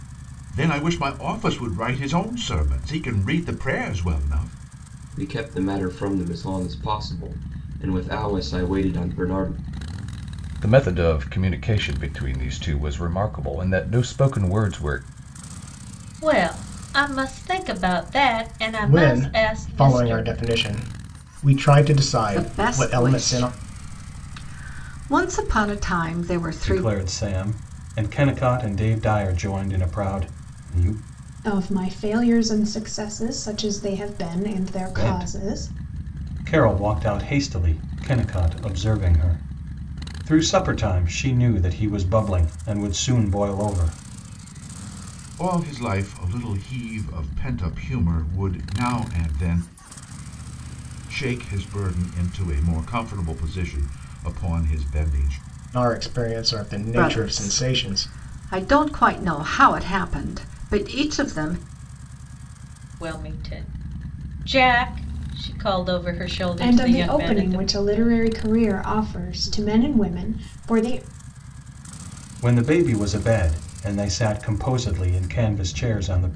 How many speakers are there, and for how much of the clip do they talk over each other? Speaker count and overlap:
8, about 8%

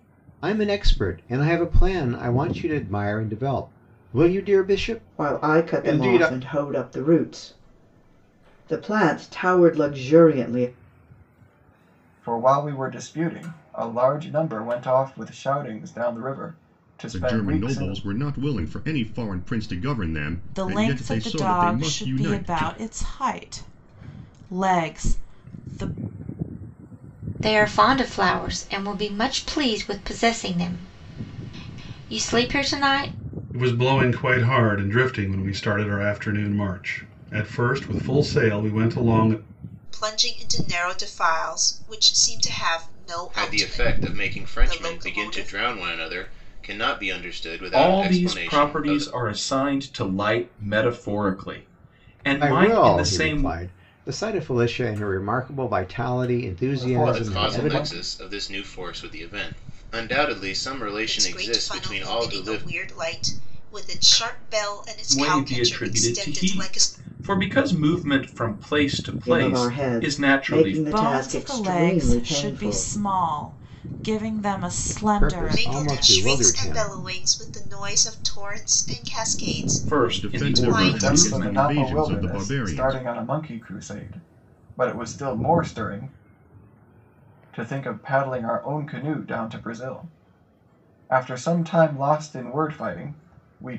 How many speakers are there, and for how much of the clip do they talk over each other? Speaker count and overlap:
10, about 24%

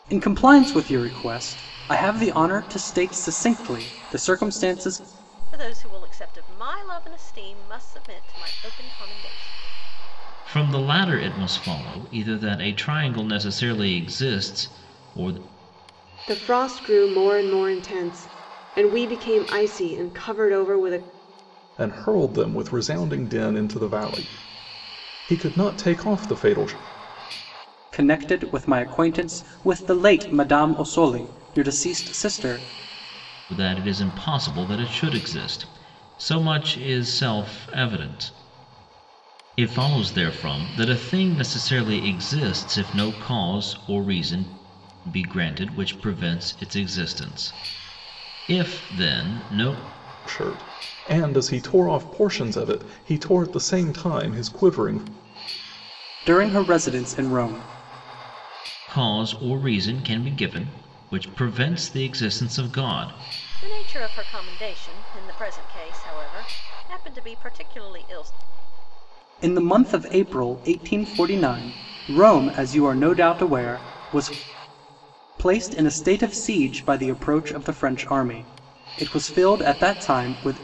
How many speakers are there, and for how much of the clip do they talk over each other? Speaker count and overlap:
5, no overlap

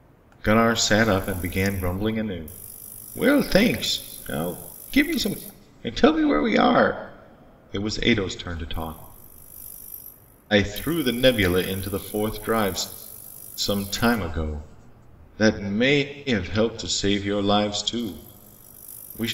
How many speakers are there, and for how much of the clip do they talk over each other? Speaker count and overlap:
1, no overlap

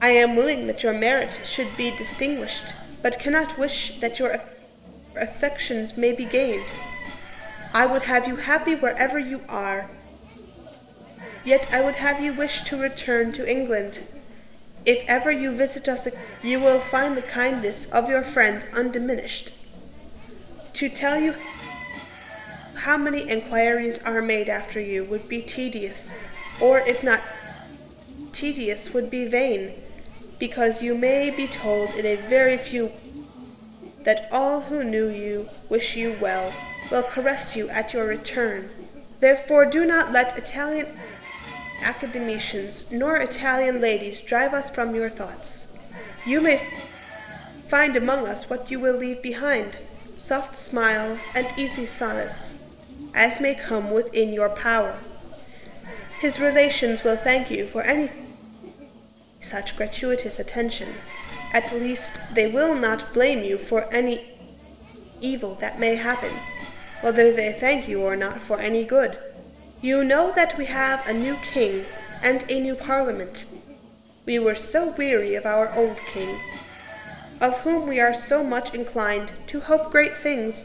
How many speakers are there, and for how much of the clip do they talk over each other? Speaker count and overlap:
1, no overlap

